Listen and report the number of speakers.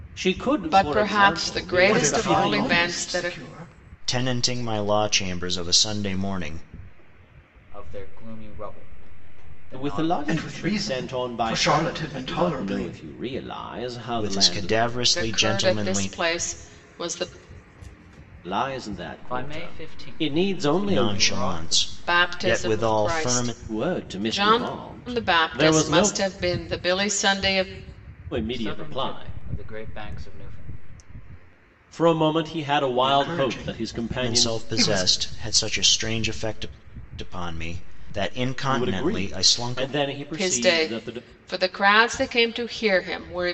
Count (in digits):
5